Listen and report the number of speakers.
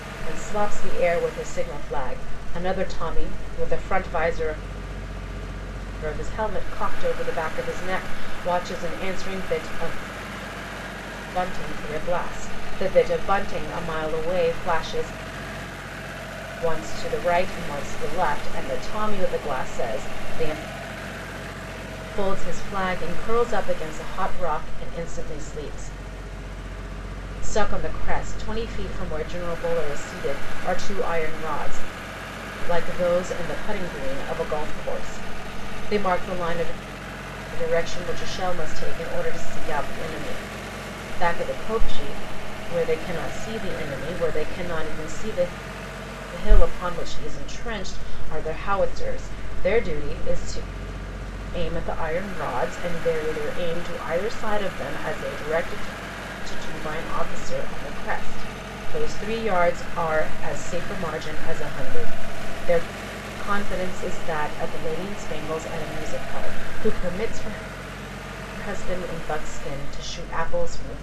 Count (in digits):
1